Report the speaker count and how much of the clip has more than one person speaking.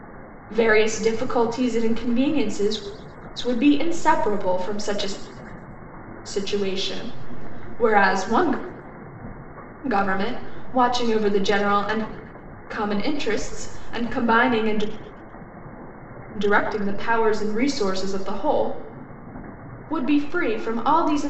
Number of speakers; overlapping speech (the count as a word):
one, no overlap